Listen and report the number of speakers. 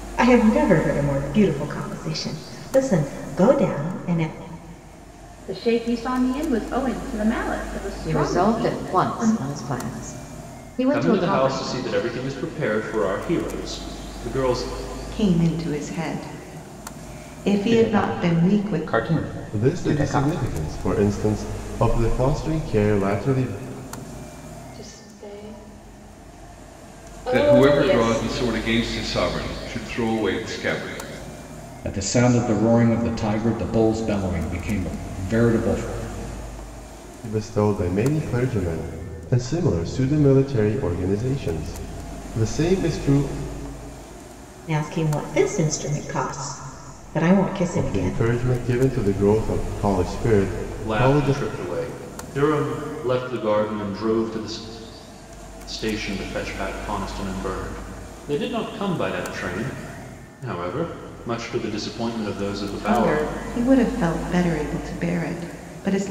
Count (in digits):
10